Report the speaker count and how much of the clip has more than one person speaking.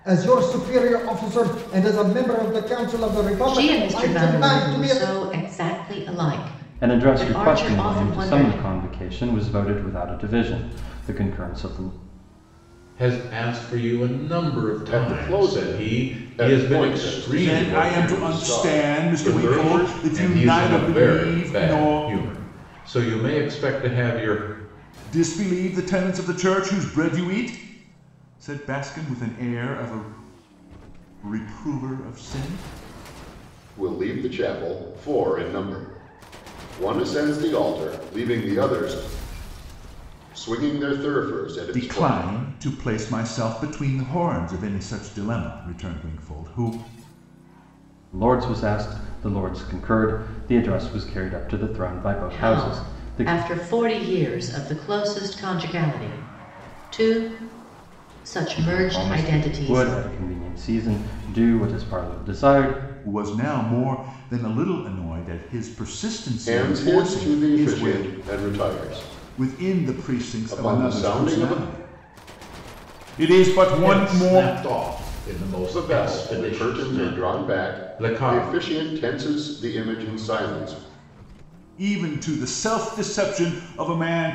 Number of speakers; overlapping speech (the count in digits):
6, about 25%